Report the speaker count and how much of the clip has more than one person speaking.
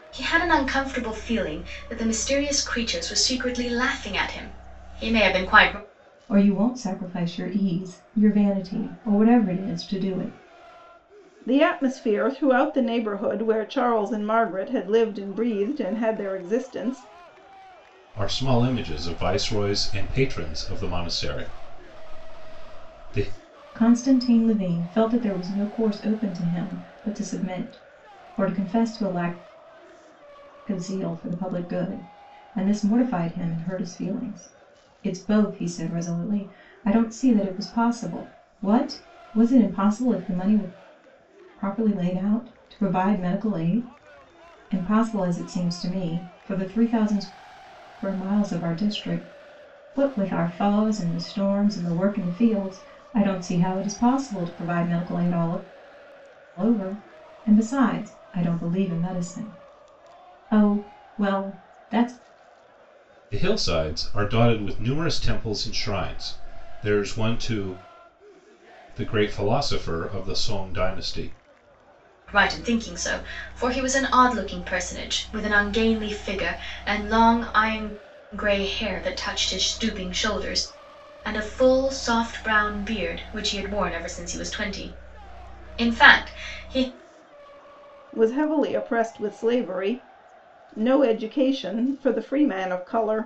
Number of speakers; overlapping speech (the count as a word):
four, no overlap